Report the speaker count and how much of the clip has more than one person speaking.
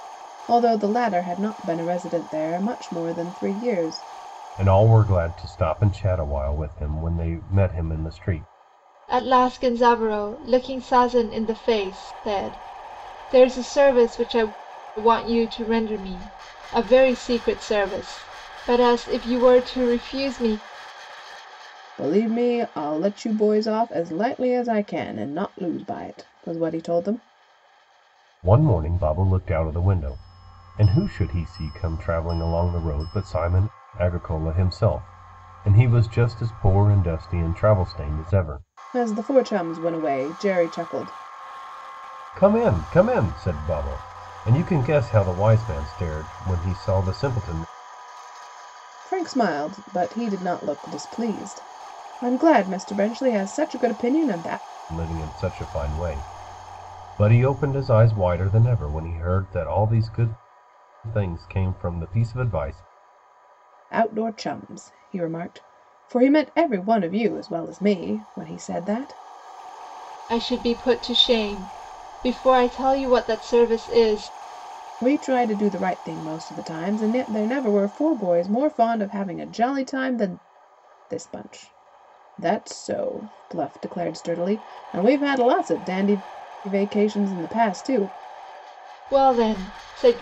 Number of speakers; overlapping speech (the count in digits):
3, no overlap